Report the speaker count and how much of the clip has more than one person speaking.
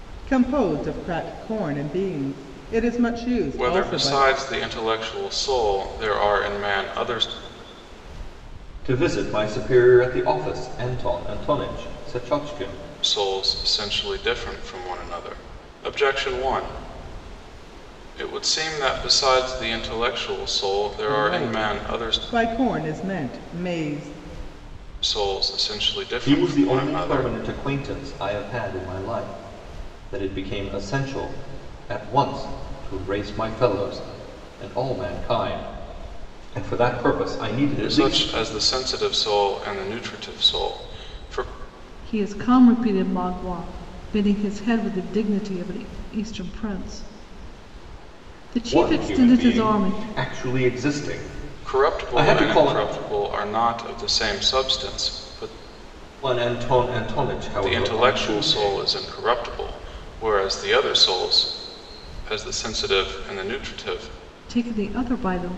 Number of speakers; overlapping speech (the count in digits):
3, about 11%